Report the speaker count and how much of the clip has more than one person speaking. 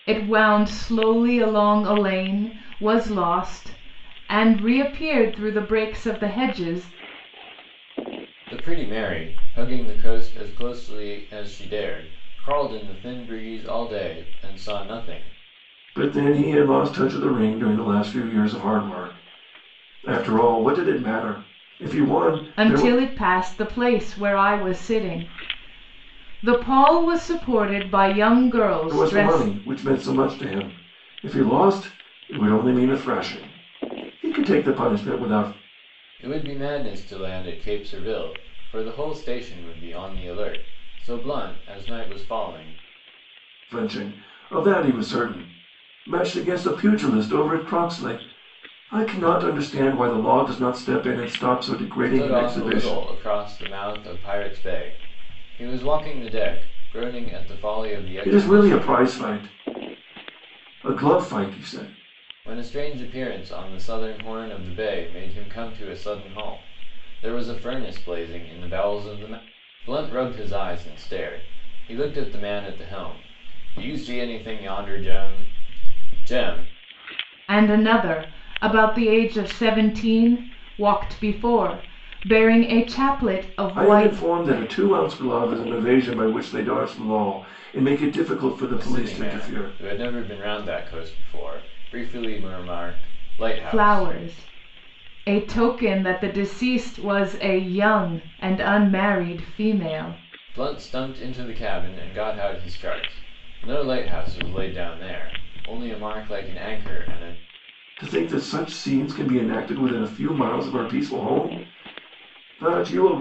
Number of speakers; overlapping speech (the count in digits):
3, about 4%